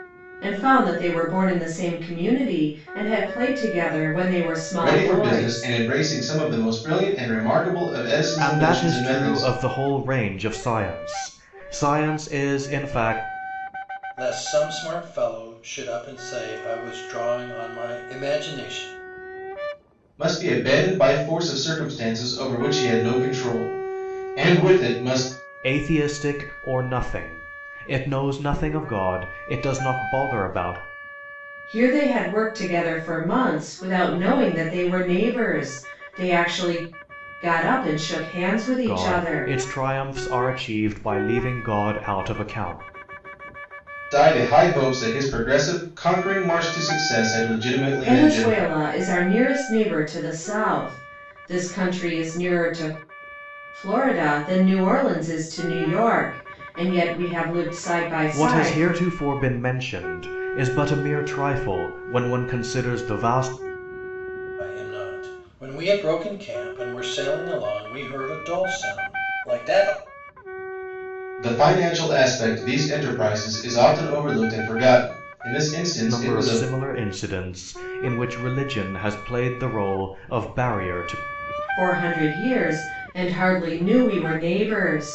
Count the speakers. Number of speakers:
4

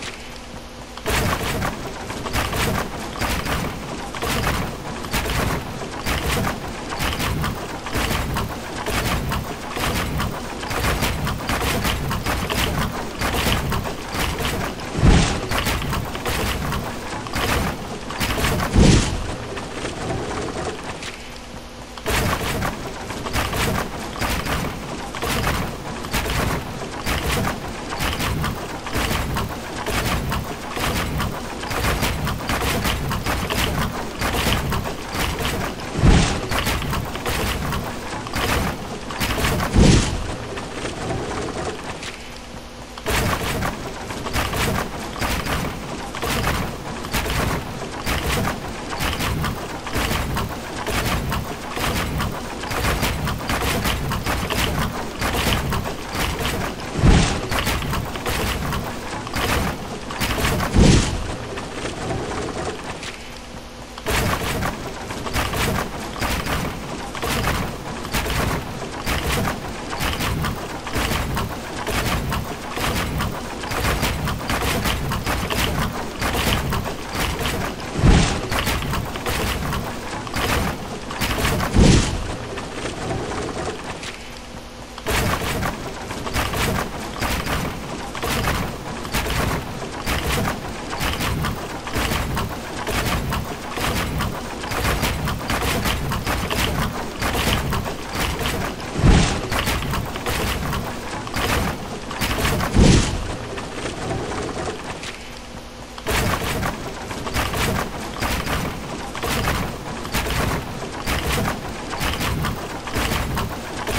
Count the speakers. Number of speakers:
0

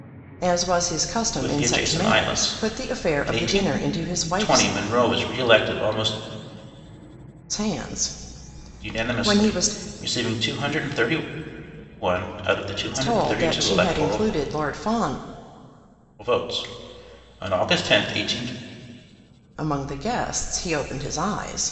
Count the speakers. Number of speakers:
2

